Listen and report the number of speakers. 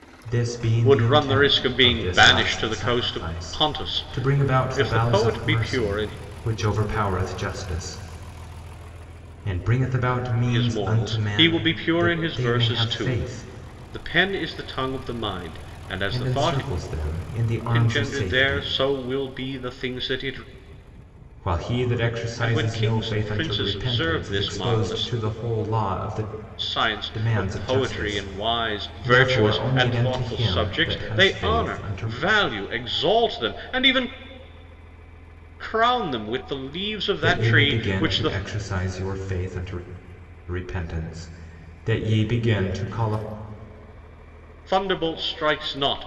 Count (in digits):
2